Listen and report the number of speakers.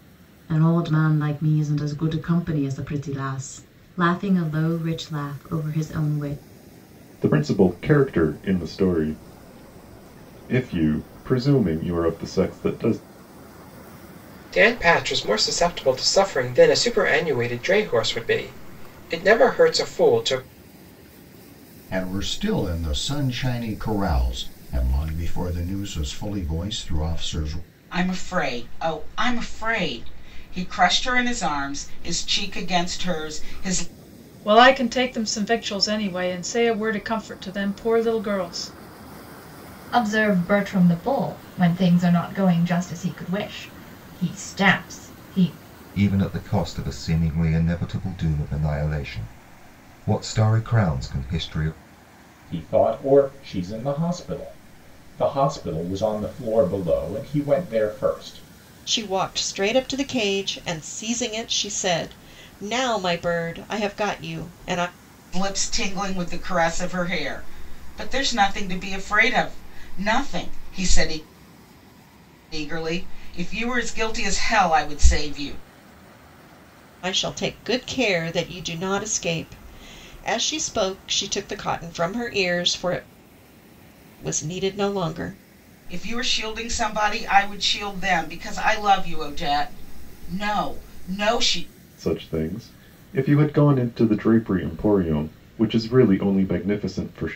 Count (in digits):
10